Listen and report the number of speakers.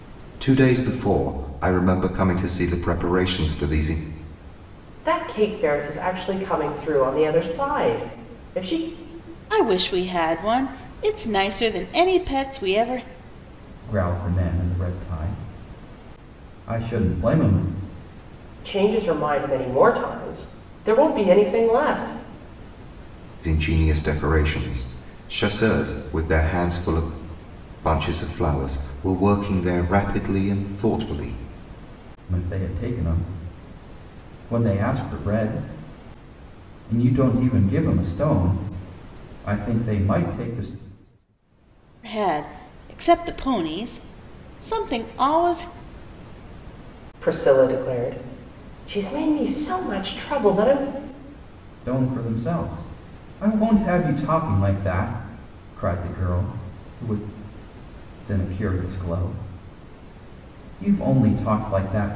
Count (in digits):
4